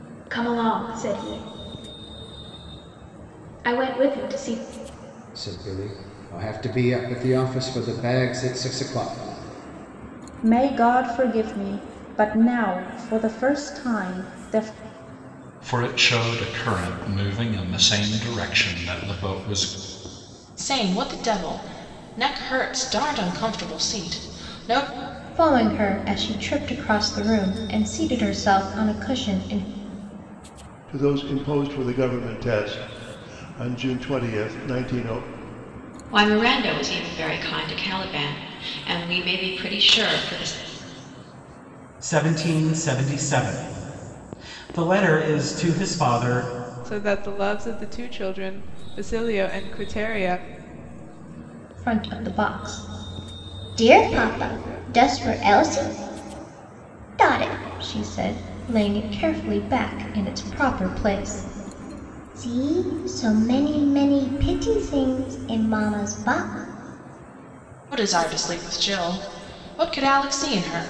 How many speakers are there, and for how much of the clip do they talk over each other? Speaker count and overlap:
10, no overlap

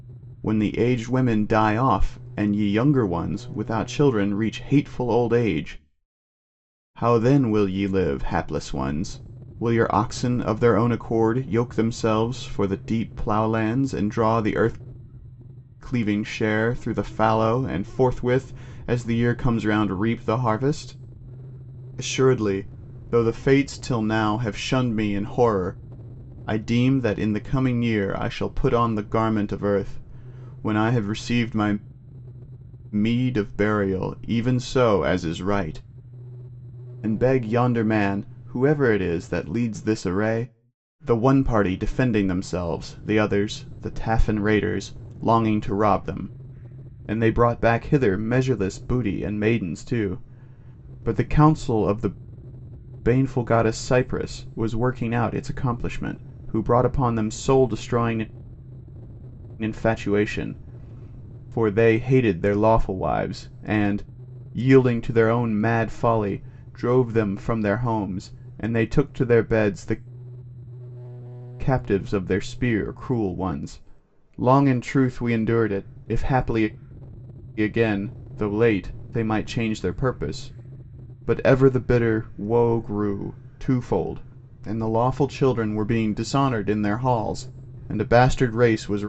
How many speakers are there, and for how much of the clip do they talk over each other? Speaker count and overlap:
1, no overlap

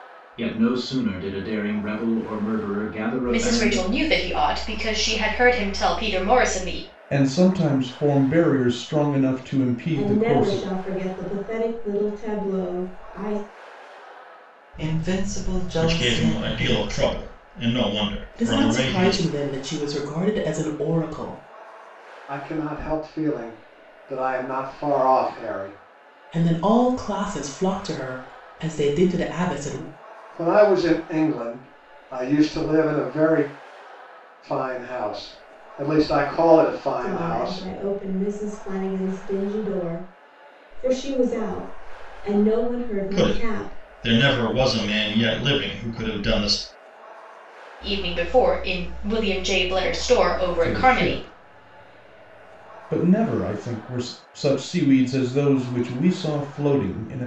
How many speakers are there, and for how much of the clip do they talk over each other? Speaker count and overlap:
8, about 10%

